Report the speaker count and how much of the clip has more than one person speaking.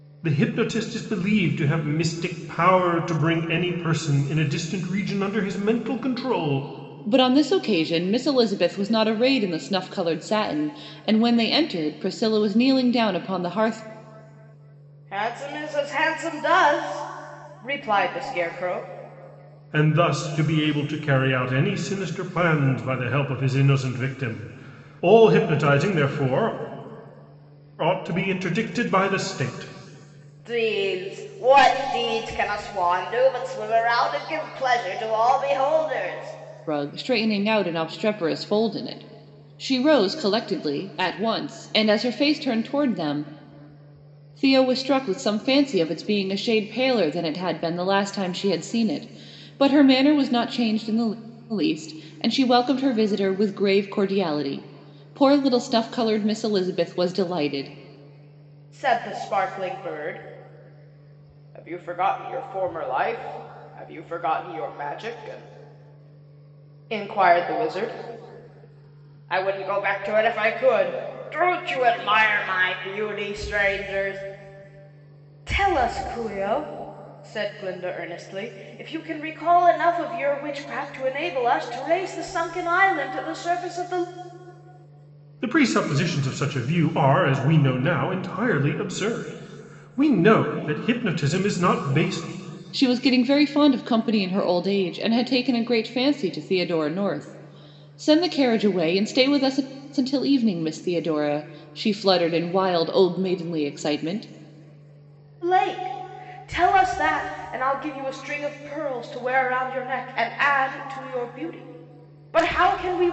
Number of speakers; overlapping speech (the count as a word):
three, no overlap